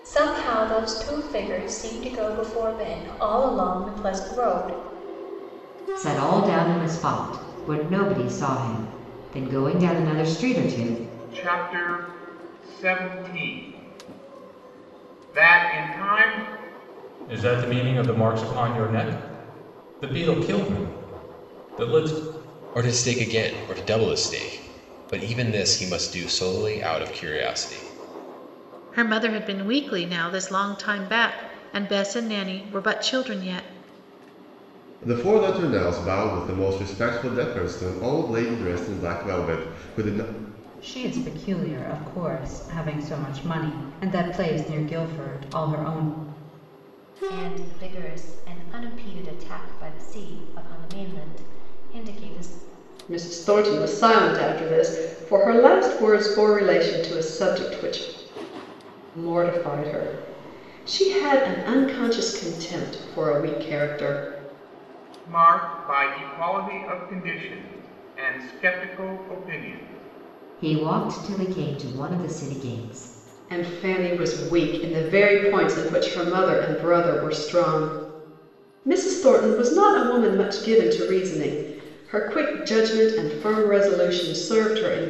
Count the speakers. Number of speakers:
ten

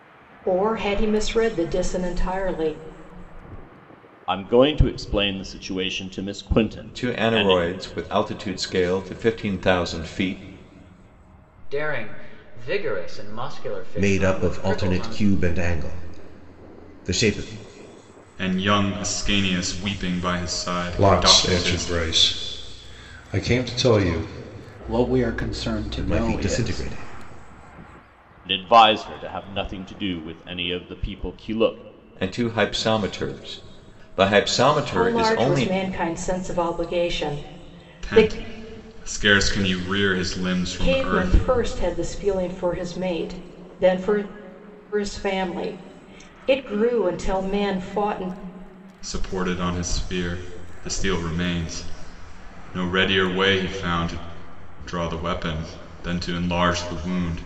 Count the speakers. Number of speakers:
eight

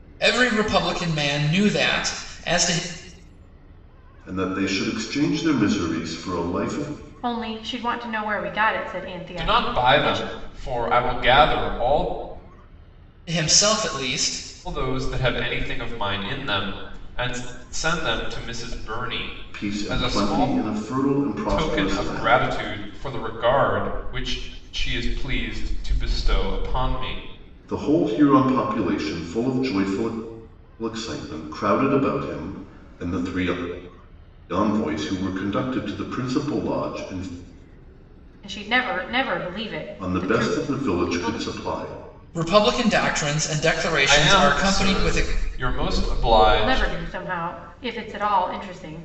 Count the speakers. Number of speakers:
four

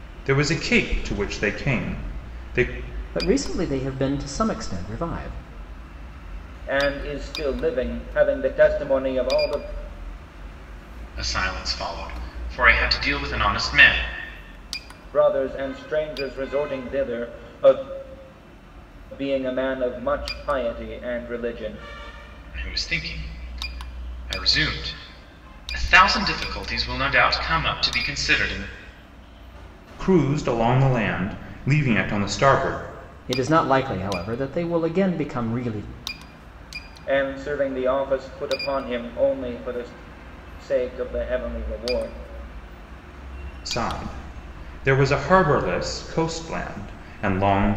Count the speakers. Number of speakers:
four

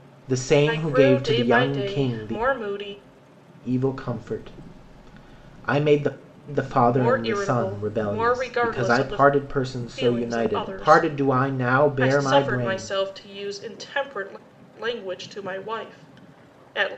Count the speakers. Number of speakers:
two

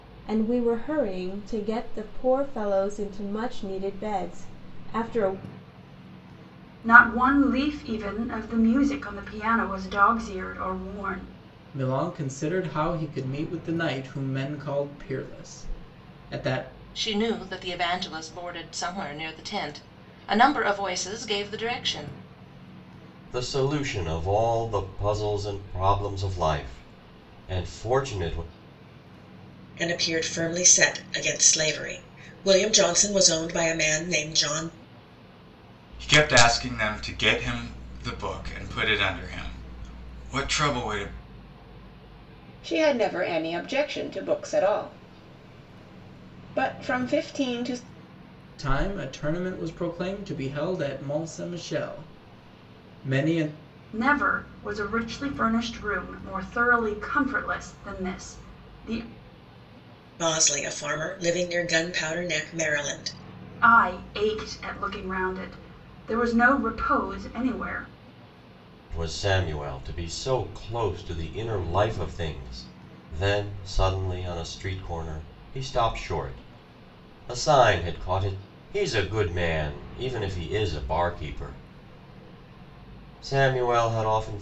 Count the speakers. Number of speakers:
eight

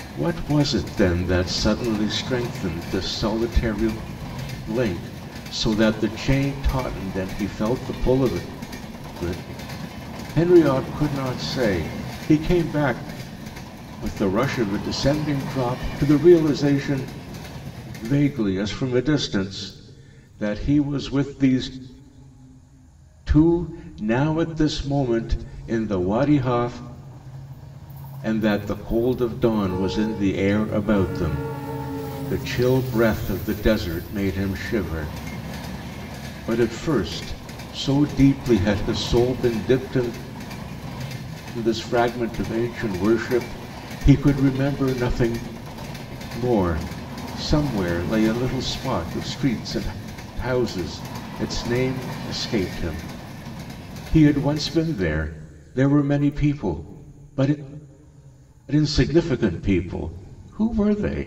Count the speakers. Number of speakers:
one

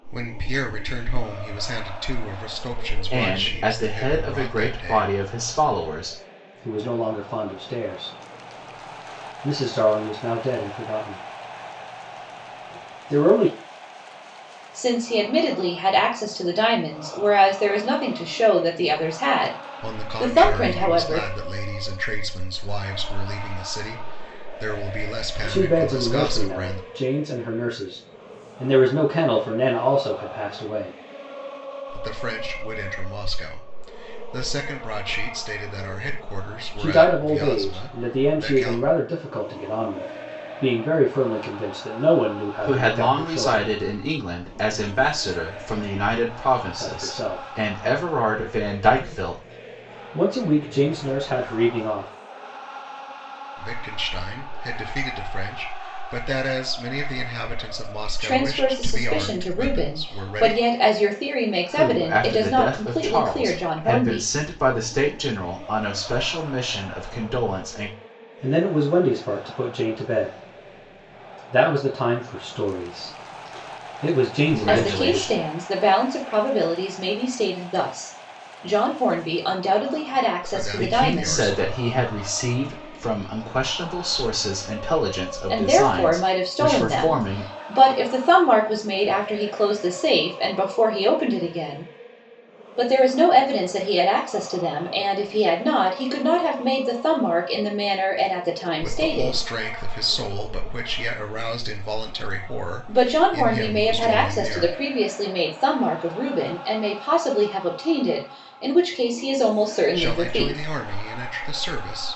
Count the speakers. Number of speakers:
four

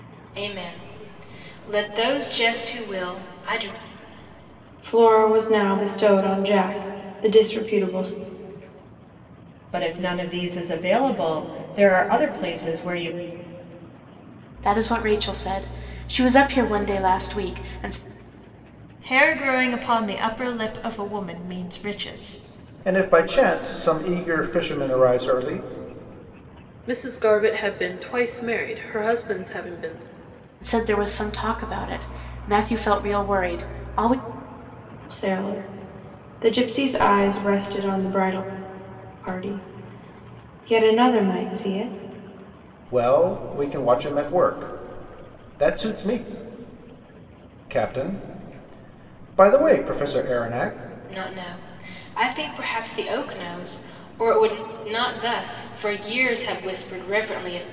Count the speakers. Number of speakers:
seven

